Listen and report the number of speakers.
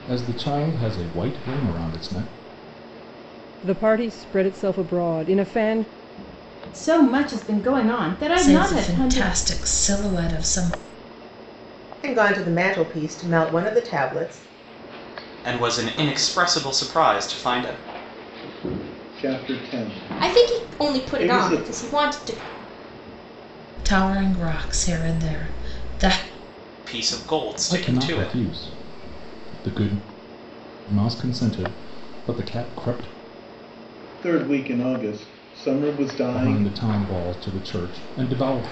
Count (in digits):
8